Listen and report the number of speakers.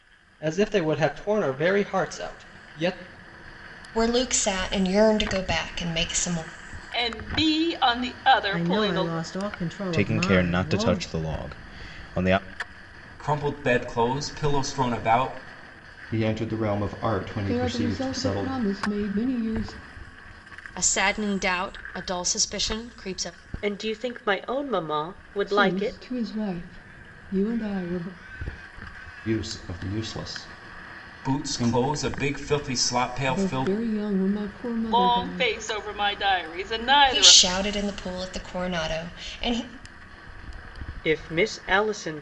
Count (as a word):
ten